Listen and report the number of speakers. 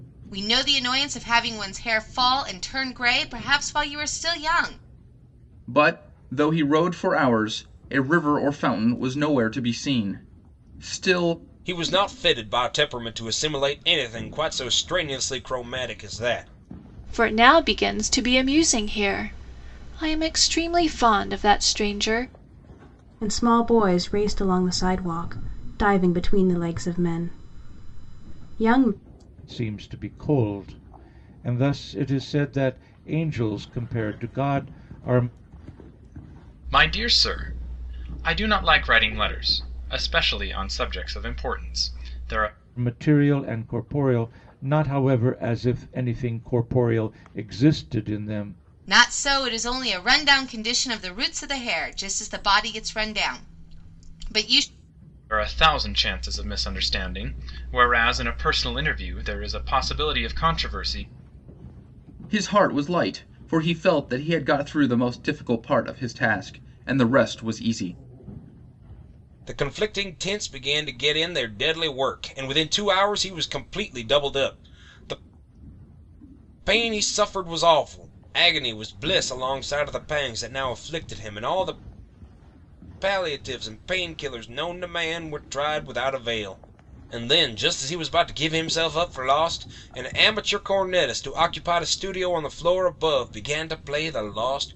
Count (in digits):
7